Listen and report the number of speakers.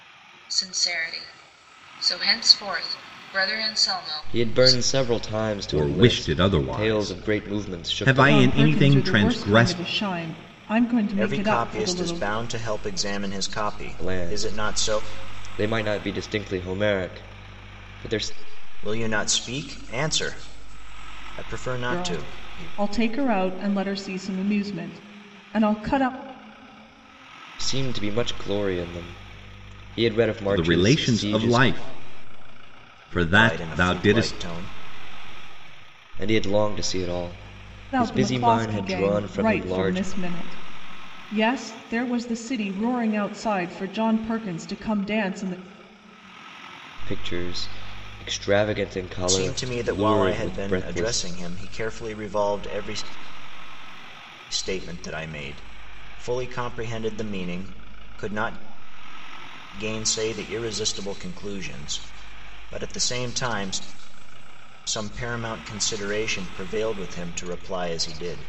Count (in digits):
5